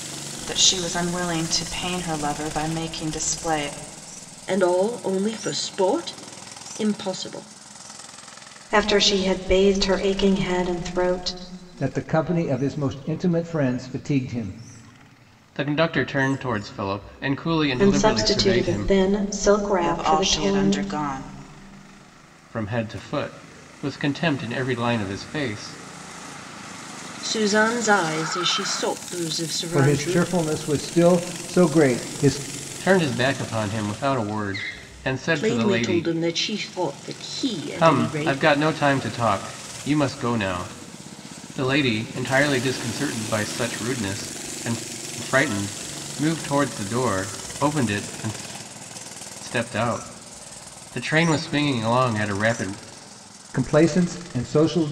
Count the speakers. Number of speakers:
5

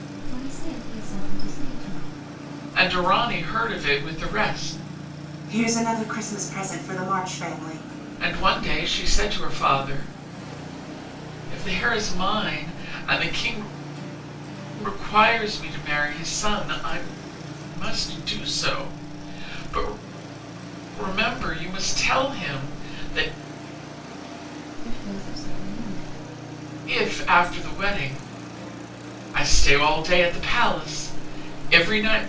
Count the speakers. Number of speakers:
3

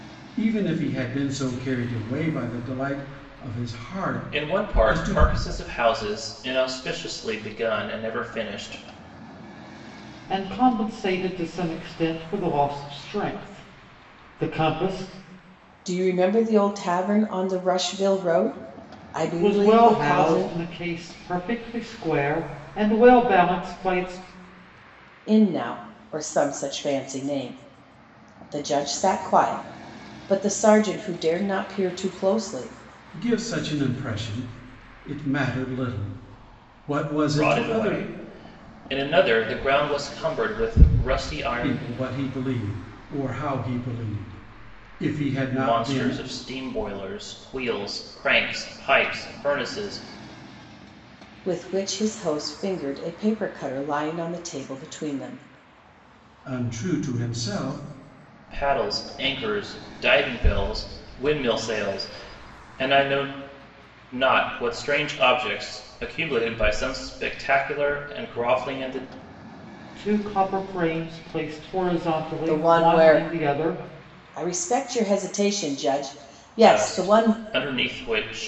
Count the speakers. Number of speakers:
4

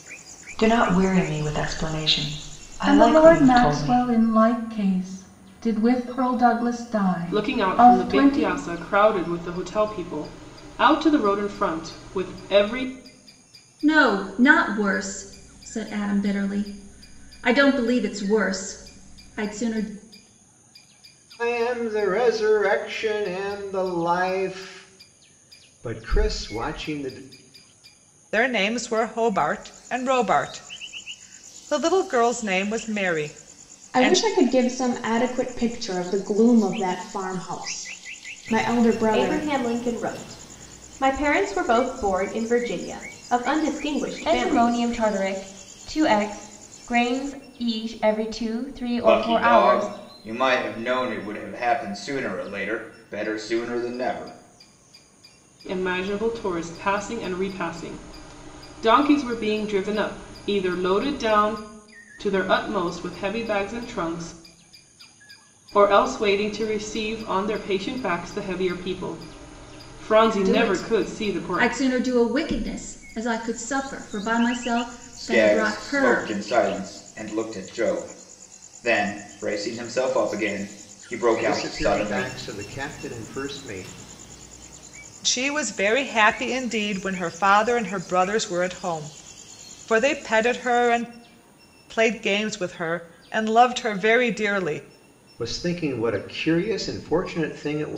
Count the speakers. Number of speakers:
10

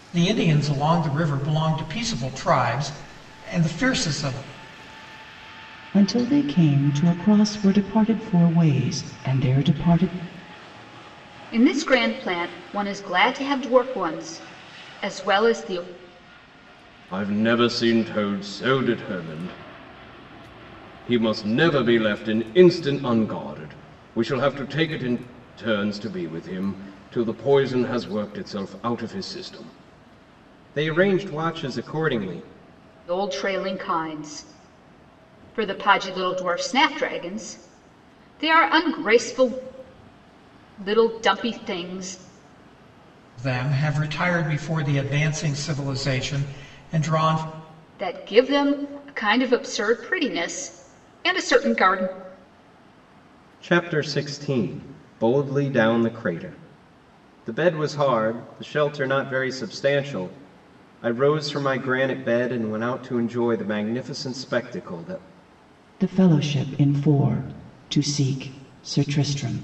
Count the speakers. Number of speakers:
4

